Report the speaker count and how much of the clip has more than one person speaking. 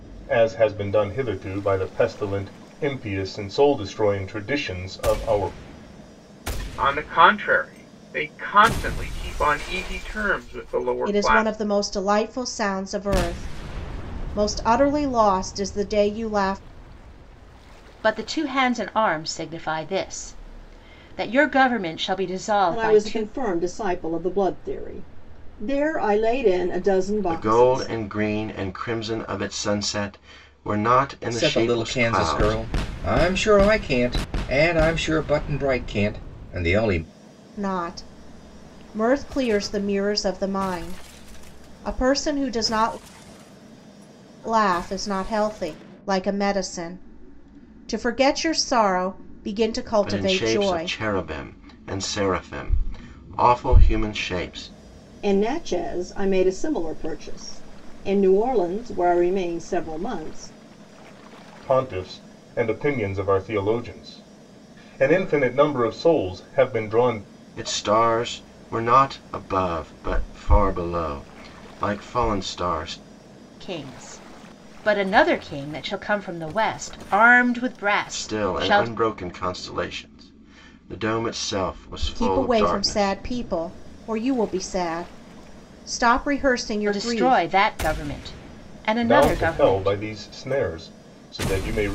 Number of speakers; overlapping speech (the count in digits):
7, about 9%